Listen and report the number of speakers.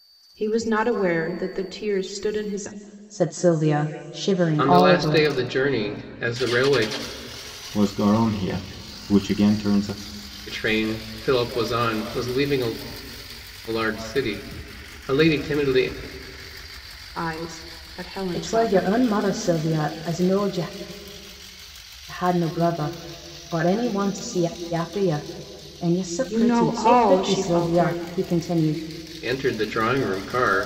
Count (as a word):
four